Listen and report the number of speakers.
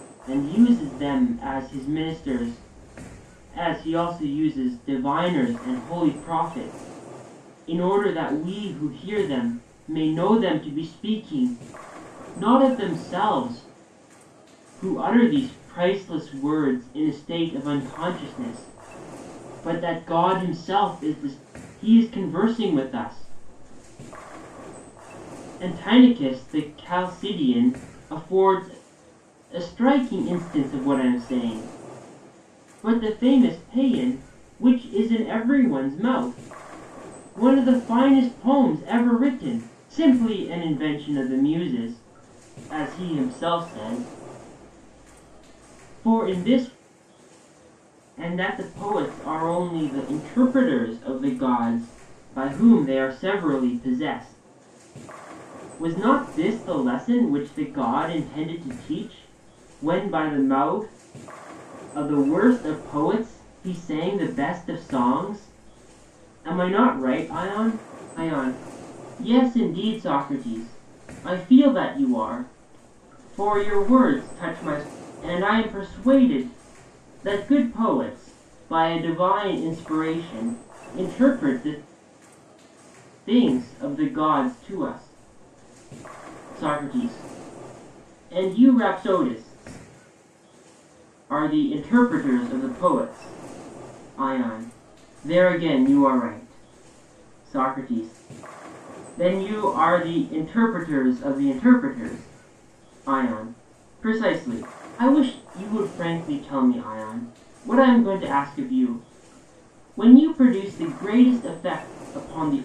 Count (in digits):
1